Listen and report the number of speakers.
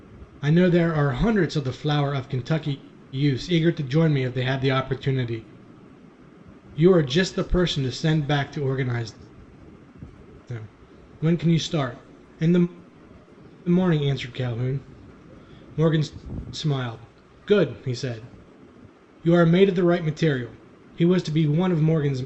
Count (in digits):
1